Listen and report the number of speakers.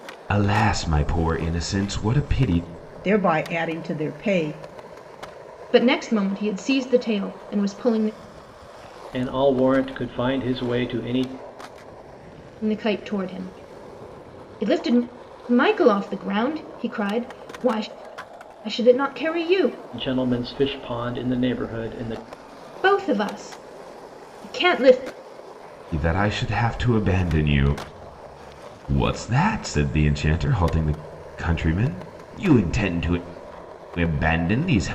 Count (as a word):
four